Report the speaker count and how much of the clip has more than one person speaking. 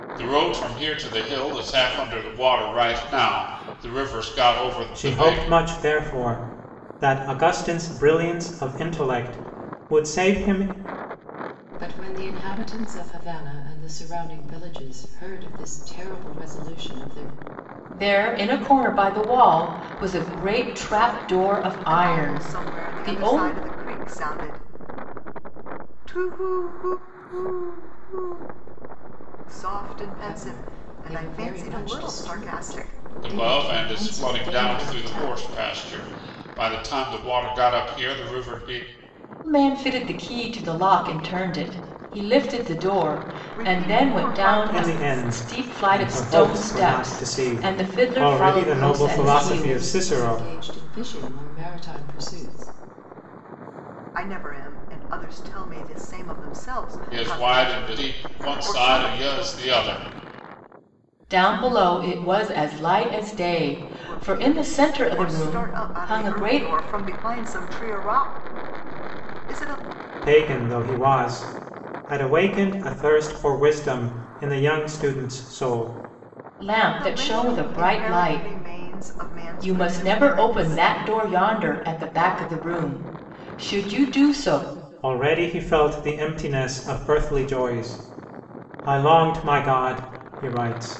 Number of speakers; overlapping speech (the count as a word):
five, about 24%